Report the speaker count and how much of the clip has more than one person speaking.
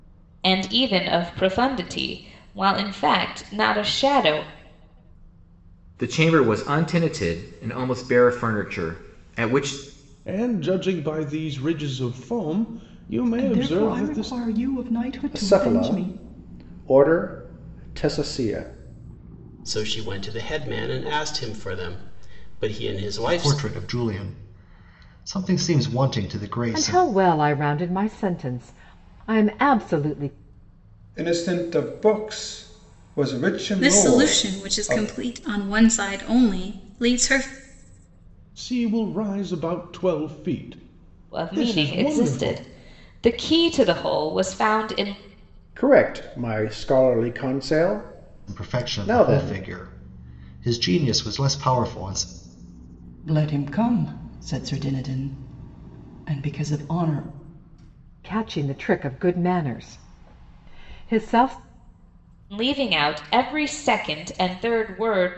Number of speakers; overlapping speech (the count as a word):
ten, about 10%